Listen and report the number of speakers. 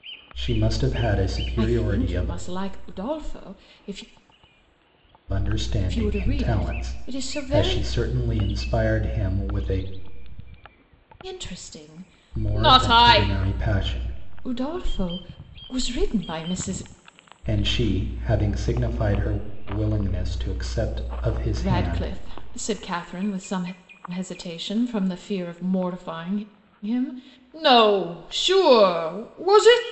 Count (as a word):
two